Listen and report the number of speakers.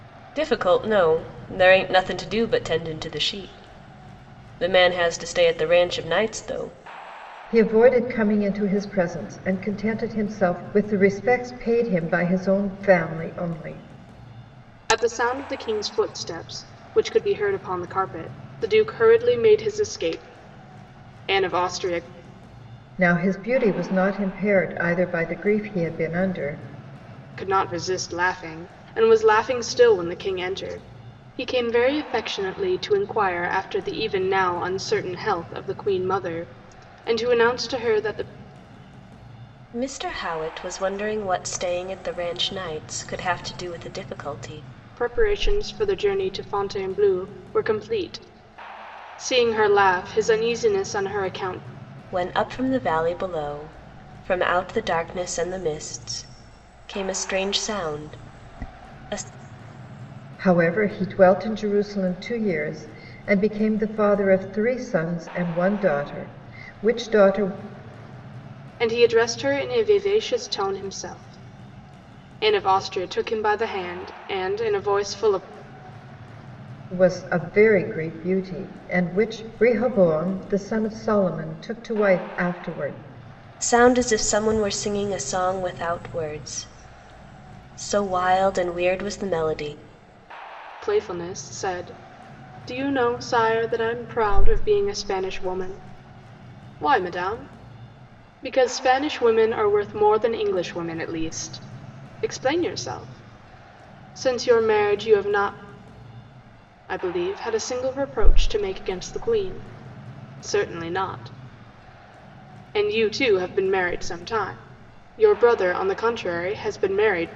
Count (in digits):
3